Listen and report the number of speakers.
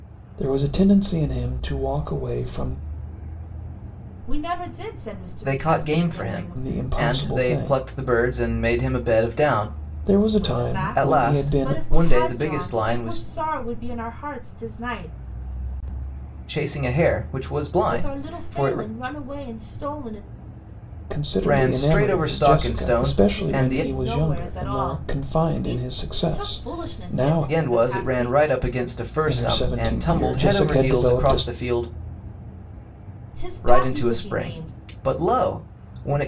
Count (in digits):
3